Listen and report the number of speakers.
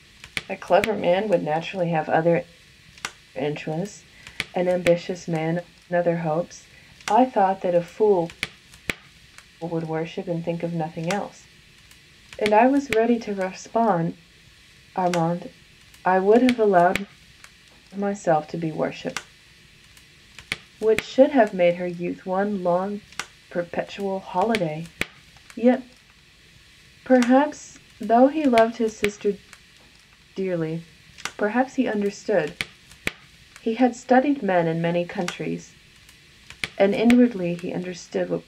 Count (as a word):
one